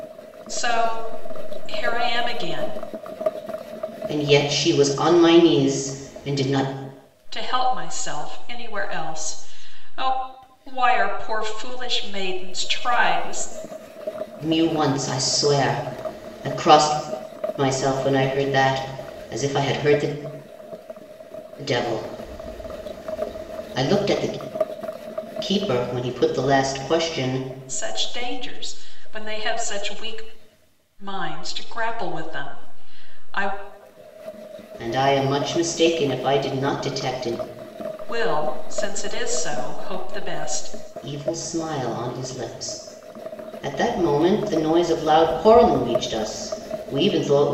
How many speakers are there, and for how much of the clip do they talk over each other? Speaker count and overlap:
2, no overlap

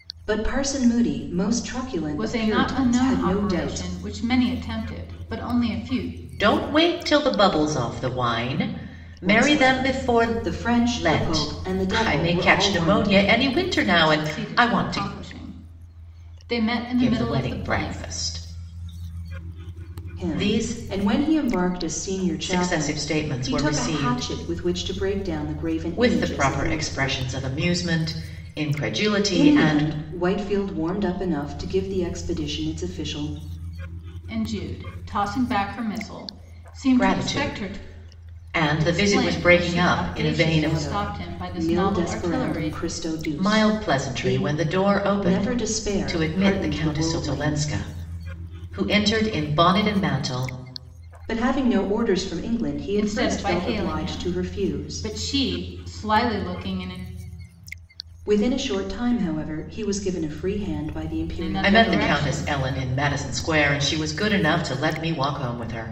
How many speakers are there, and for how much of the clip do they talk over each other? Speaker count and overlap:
3, about 36%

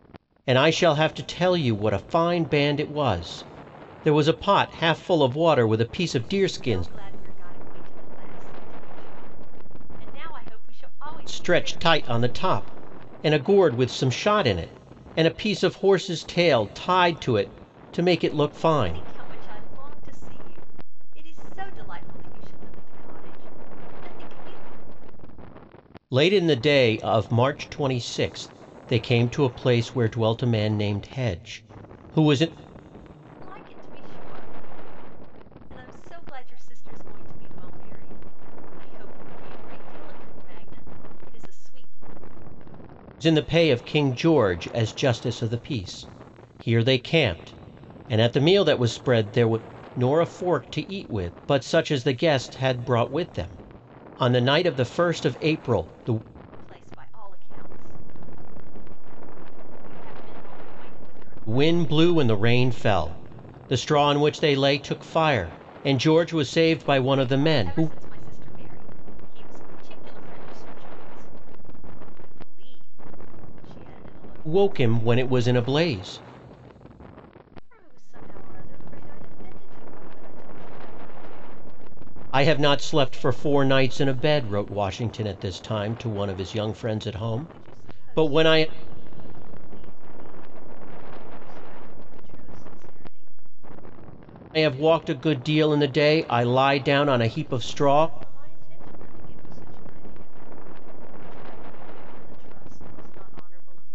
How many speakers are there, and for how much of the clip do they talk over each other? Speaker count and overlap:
2, about 9%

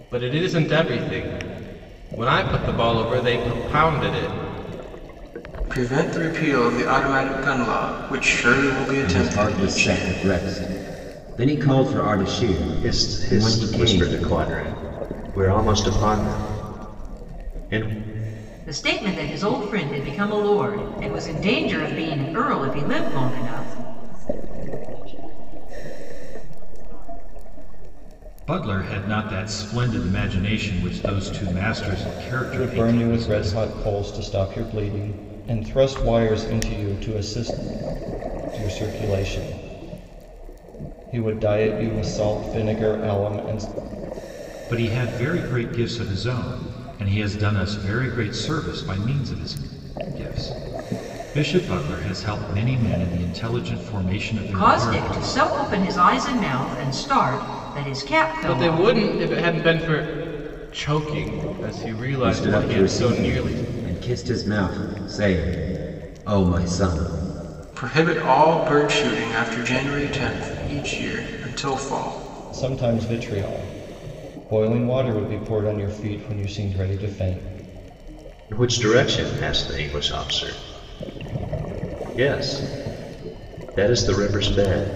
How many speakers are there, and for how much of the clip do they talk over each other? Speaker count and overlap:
8, about 9%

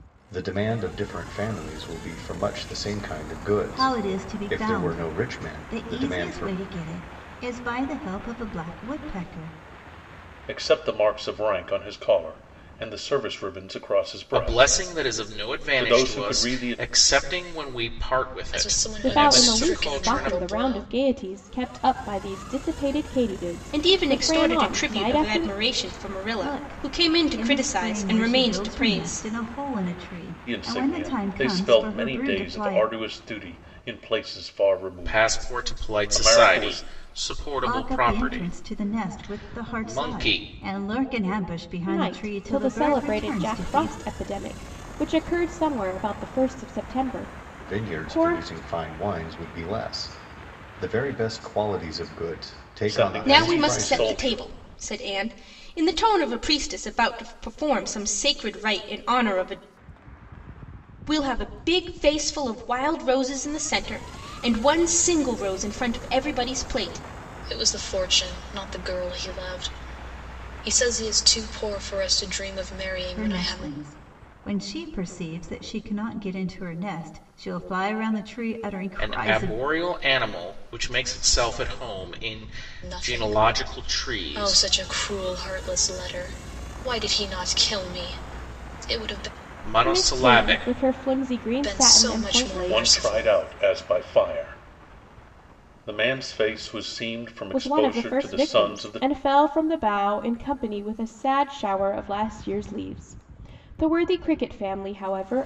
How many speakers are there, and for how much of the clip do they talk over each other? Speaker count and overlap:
7, about 30%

